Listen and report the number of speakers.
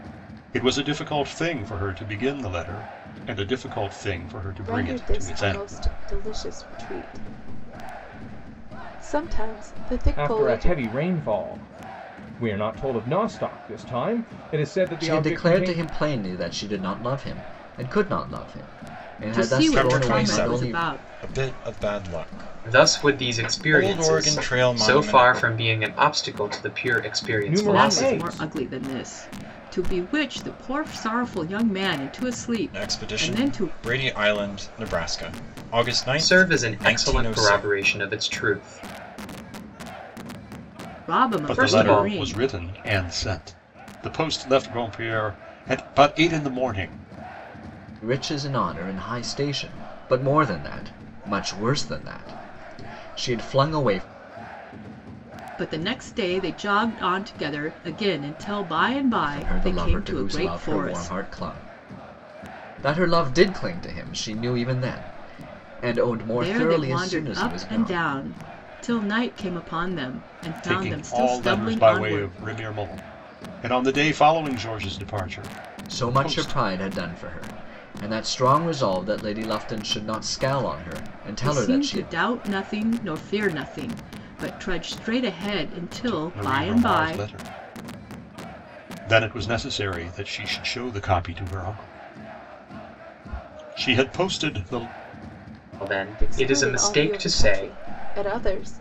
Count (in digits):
7